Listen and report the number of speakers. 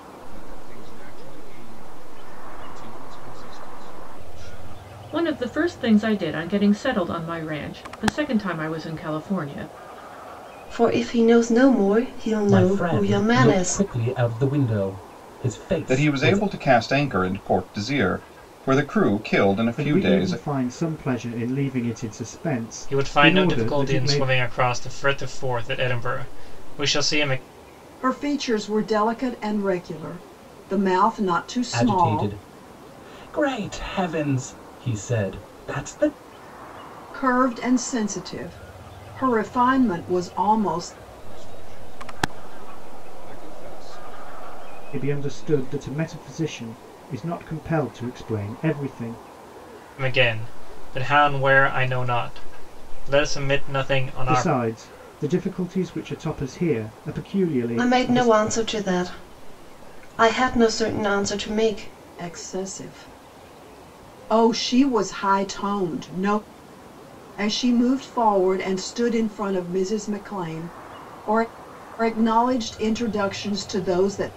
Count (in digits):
8